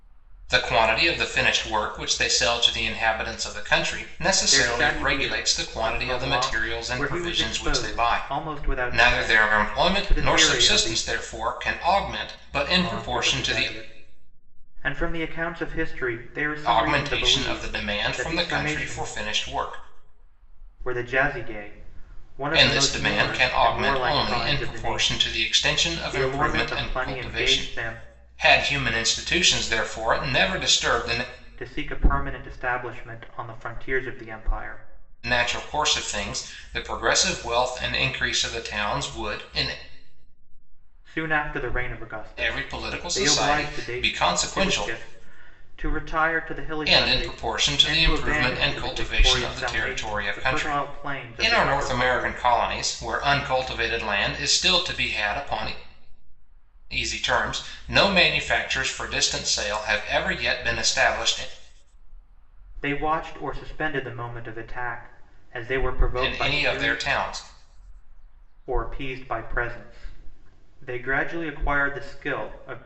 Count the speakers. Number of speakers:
two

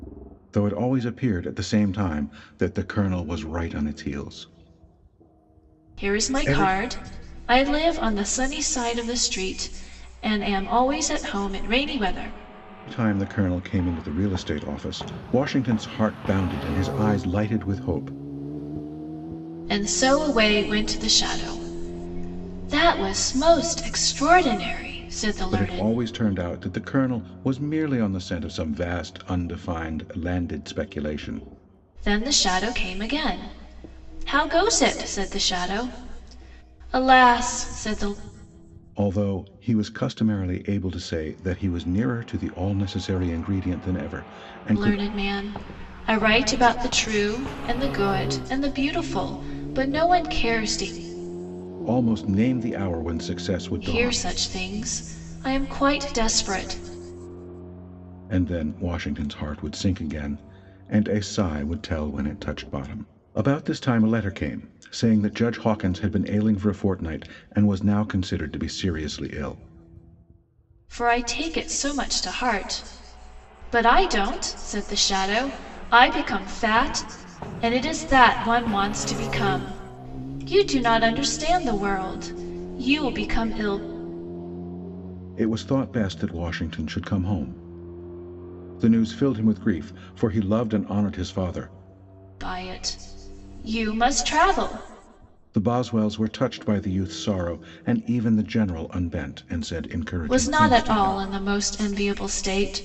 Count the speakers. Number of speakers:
two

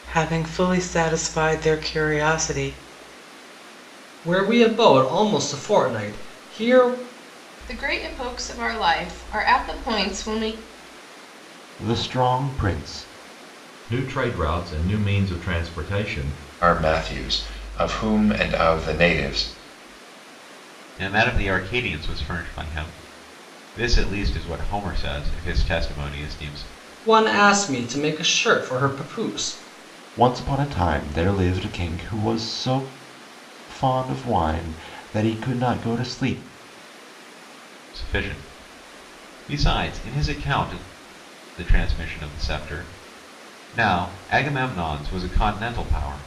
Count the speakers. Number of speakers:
seven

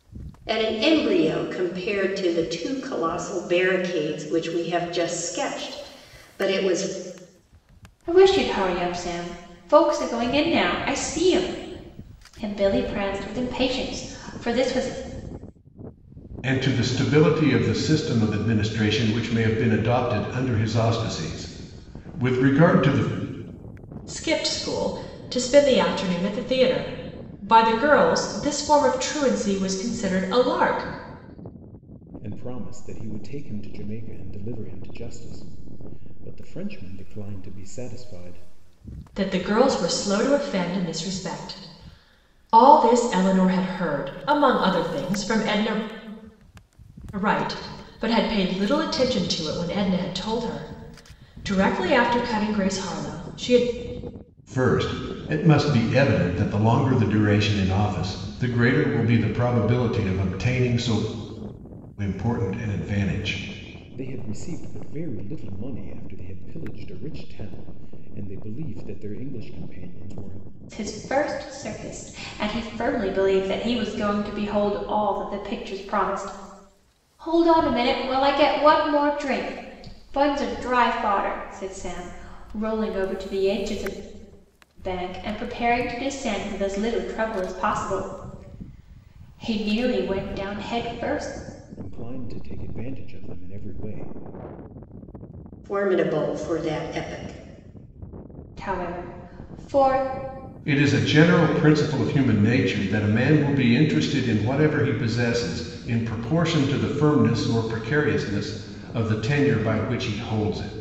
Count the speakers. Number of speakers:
five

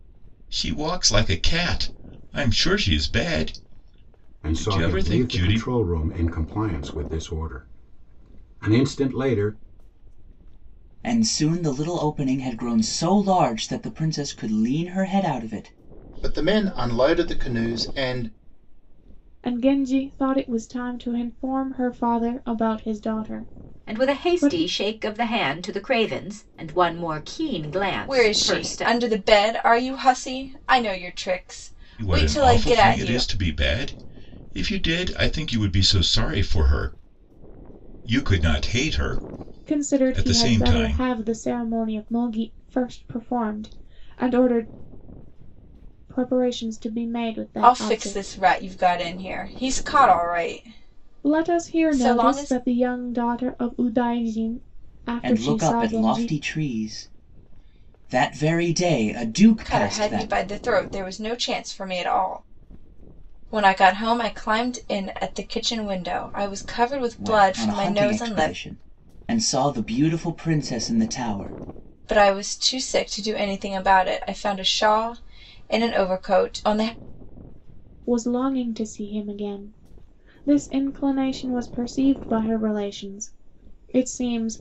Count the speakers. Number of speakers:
seven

